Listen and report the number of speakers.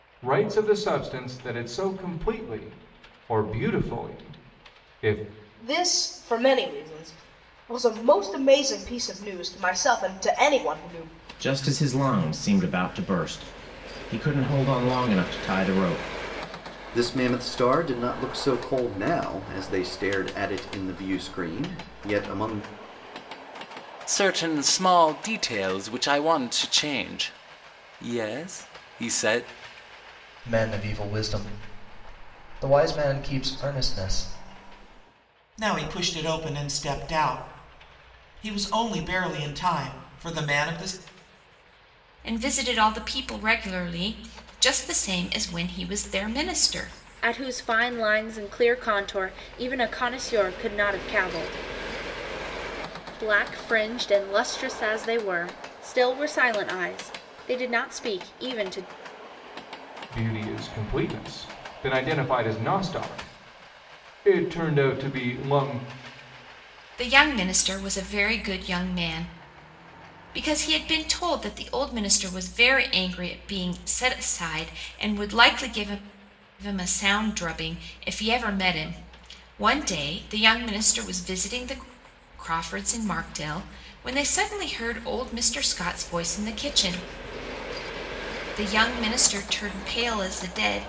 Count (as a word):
nine